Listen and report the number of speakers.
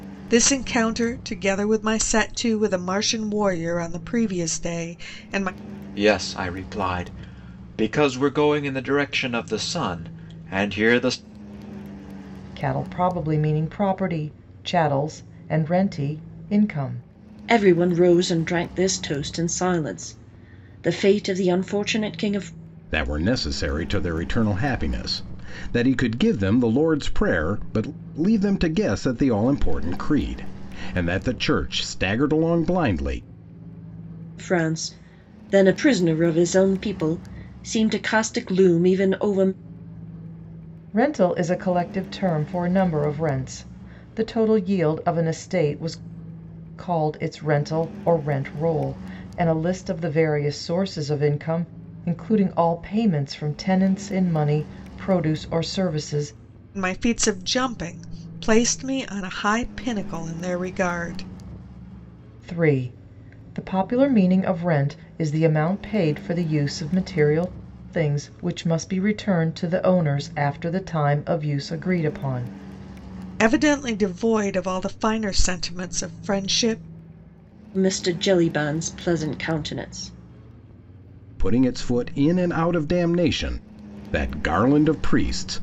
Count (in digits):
5